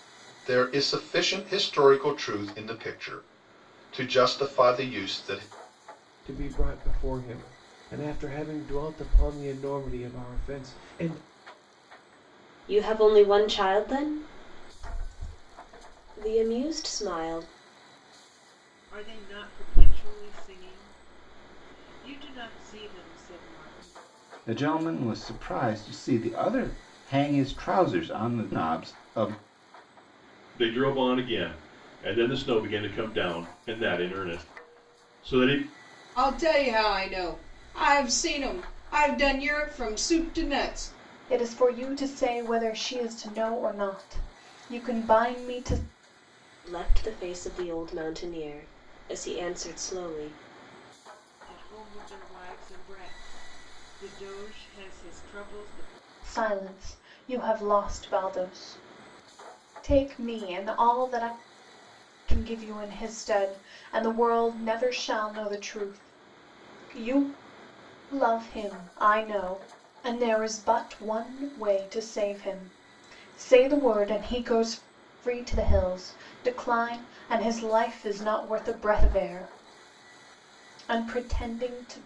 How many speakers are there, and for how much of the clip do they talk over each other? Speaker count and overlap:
8, no overlap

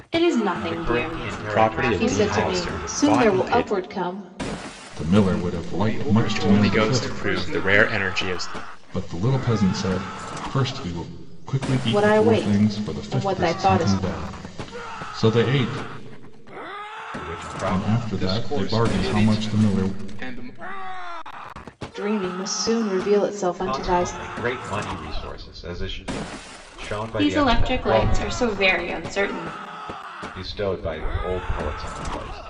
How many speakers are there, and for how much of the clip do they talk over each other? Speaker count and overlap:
6, about 37%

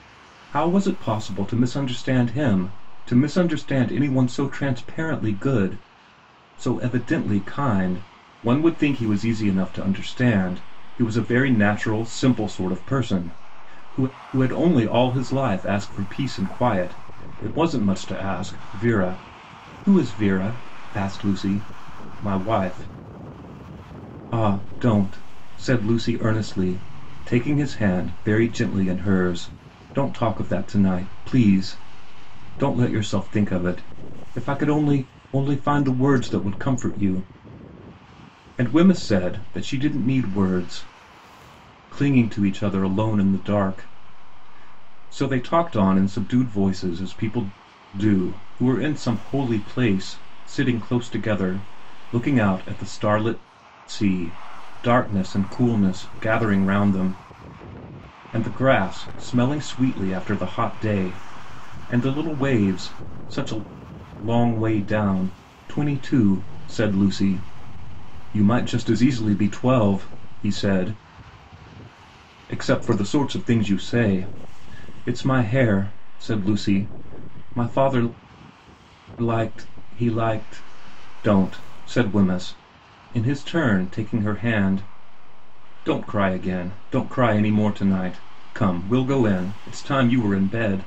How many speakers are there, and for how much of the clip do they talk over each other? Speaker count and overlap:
1, no overlap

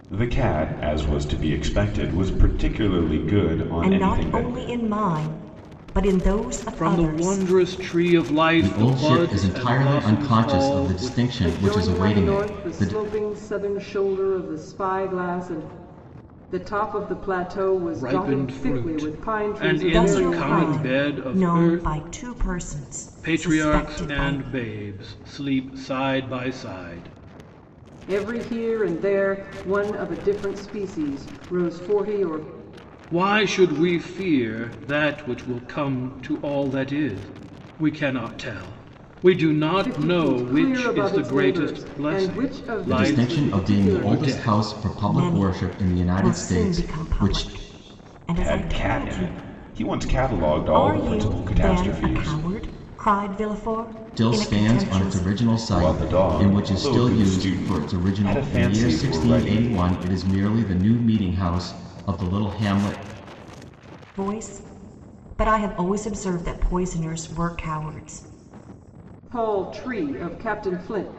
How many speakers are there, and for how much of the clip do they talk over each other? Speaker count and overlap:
5, about 37%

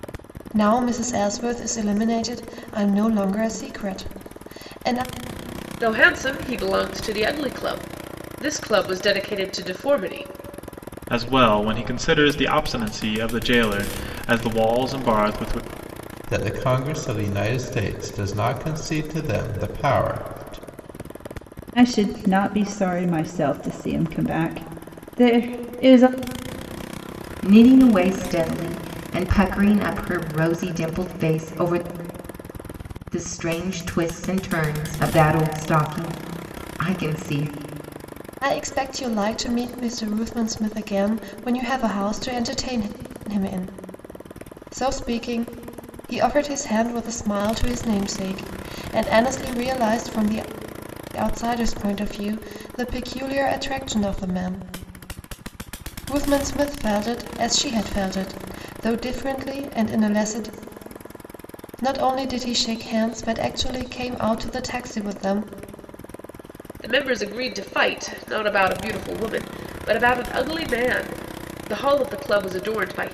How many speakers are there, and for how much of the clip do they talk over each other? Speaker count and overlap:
6, no overlap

